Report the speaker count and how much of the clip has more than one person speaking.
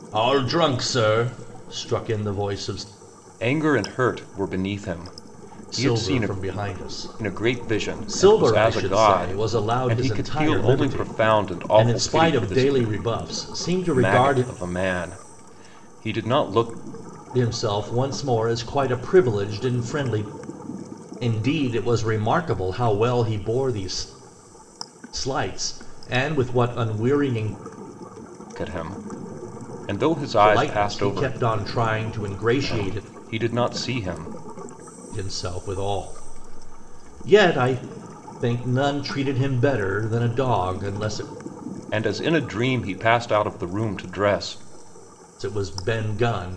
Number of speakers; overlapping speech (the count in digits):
2, about 15%